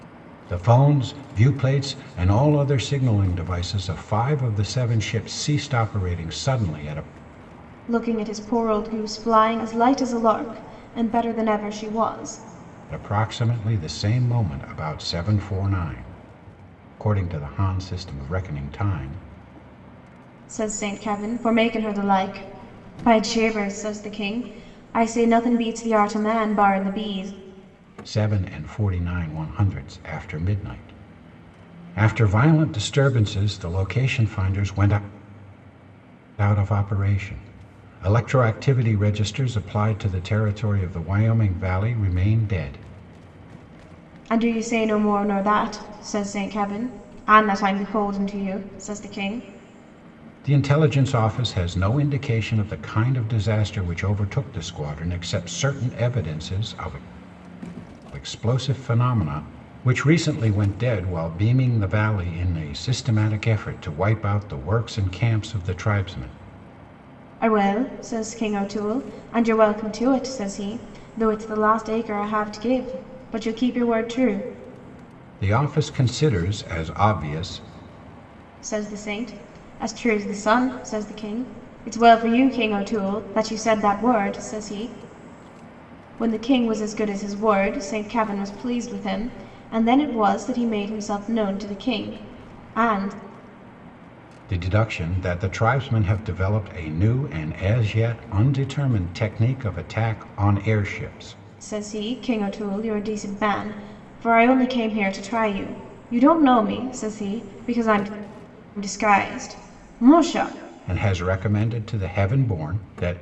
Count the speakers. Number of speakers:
two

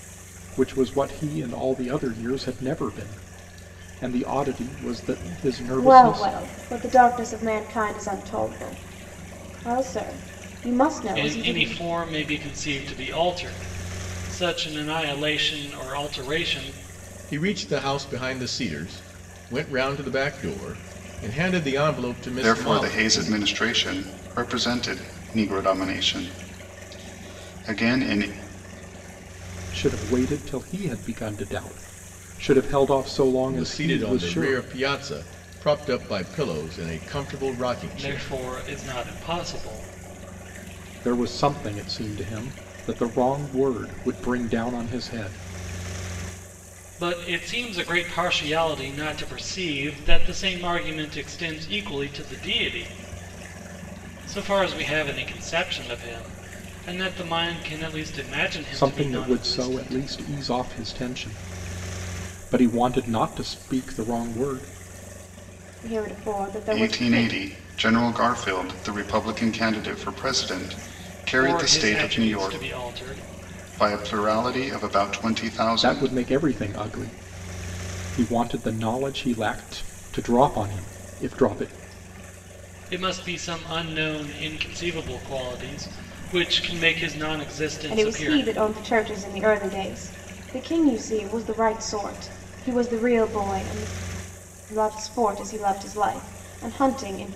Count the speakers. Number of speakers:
five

